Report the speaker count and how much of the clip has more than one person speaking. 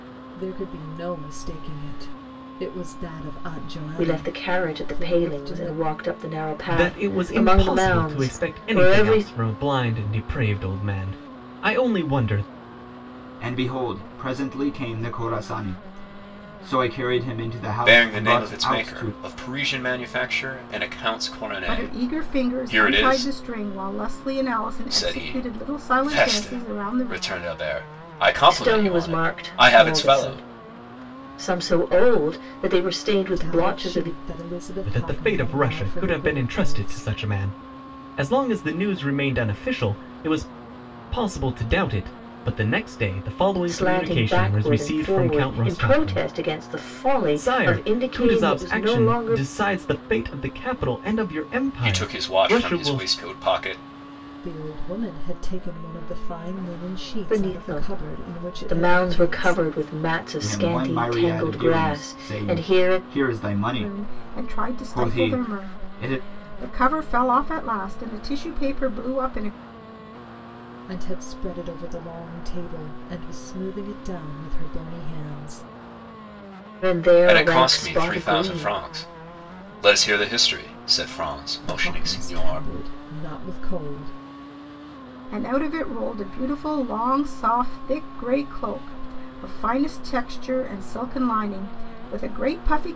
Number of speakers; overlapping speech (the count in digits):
6, about 33%